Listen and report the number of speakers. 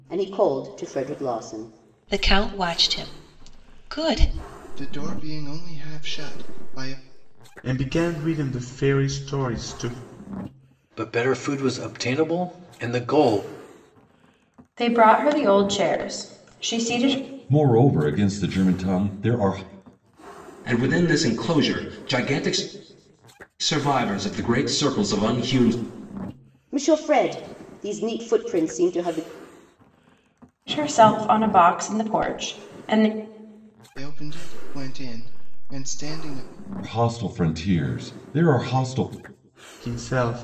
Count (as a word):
eight